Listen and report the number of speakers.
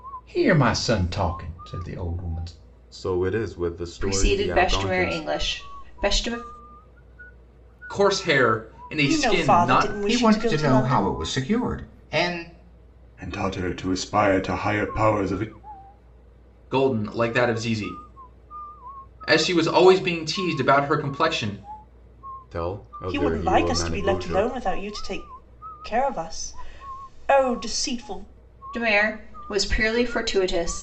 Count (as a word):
seven